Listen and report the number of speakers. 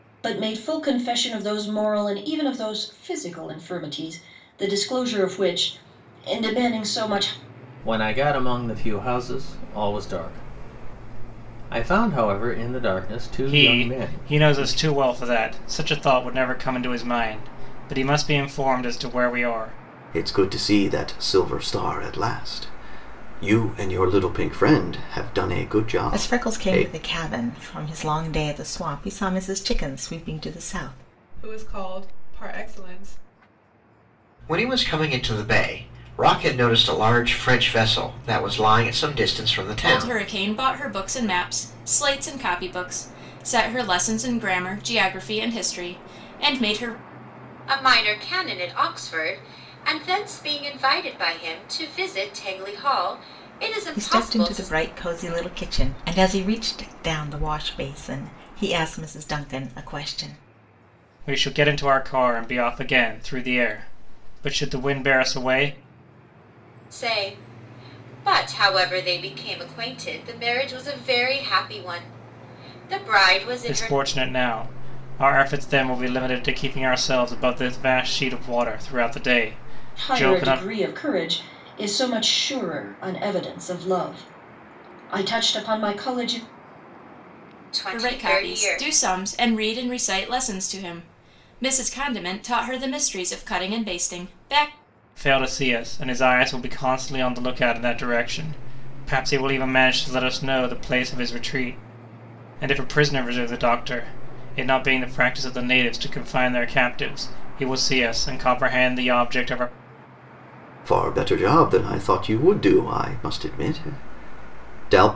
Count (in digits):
9